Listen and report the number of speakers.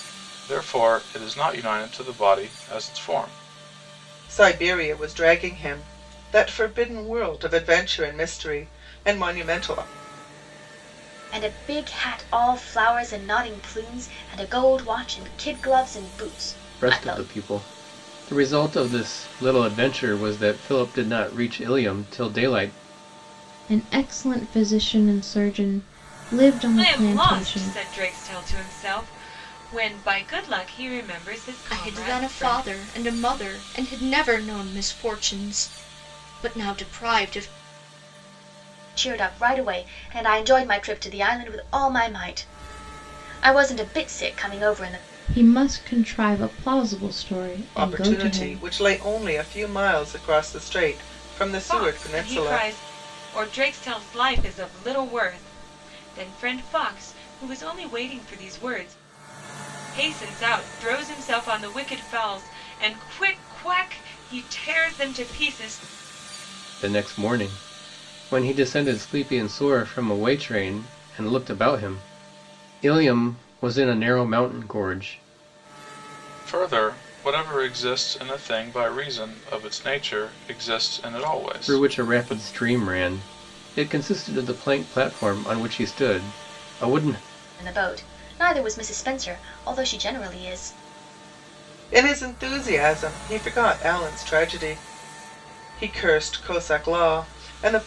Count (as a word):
seven